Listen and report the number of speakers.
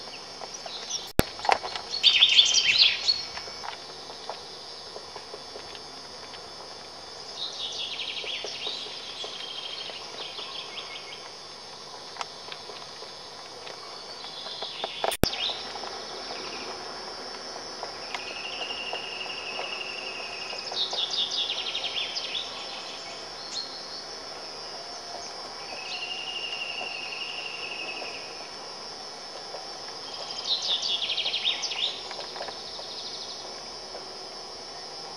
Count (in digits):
0